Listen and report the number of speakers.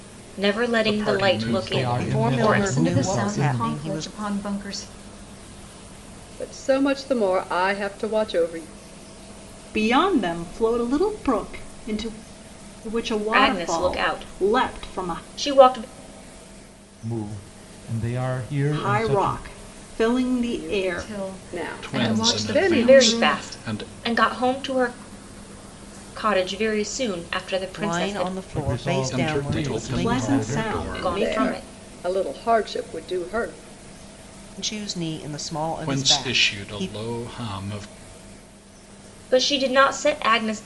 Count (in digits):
7